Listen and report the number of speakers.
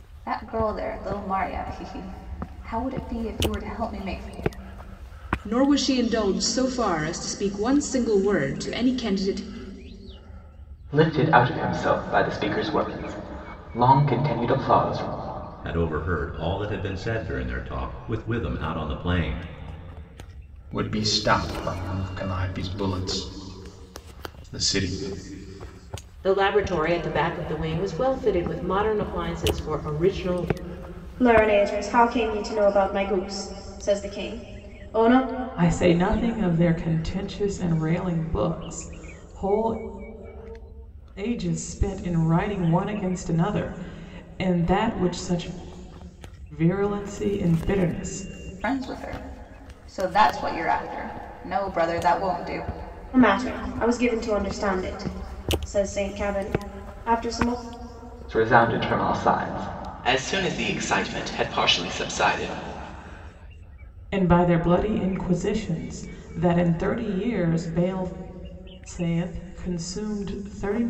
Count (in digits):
8